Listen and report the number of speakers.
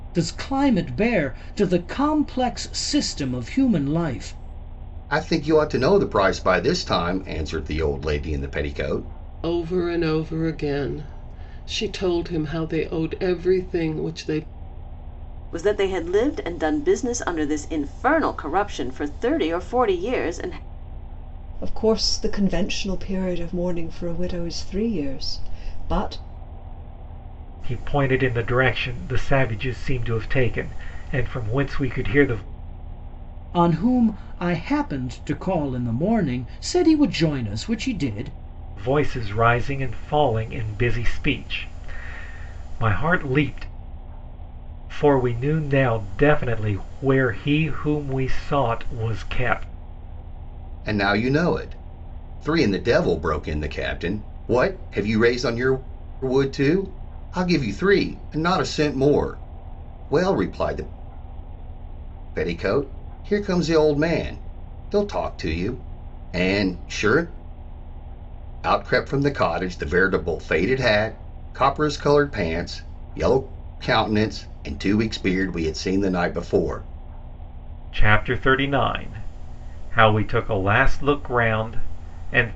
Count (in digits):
6